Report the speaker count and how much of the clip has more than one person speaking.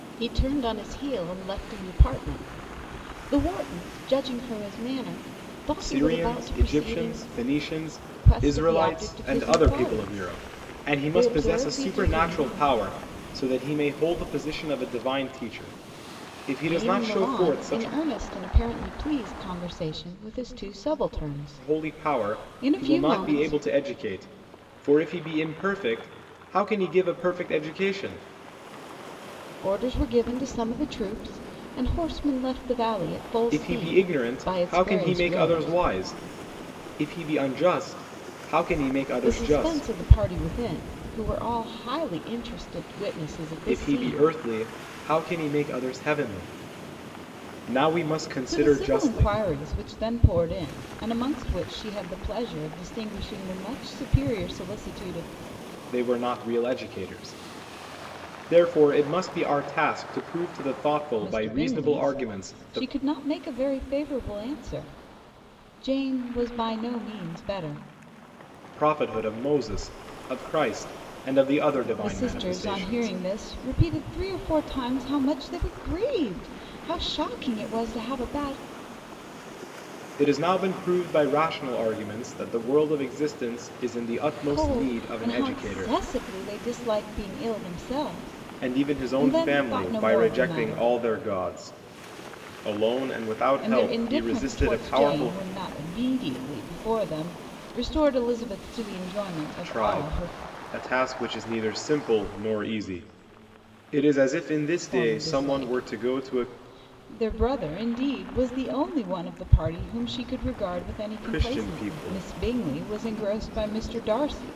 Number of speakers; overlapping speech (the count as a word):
two, about 23%